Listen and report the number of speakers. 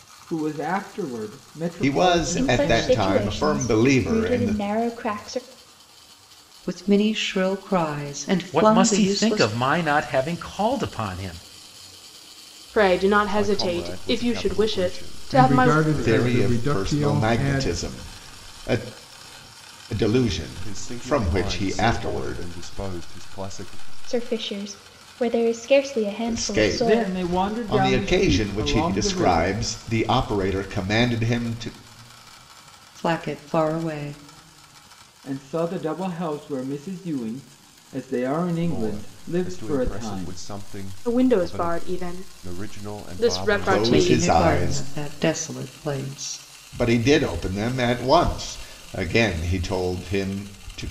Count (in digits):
8